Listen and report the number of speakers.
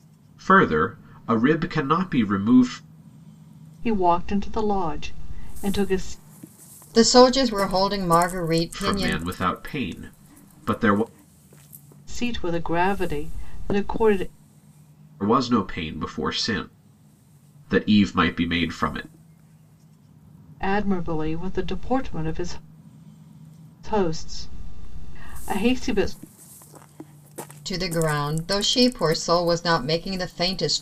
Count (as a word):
three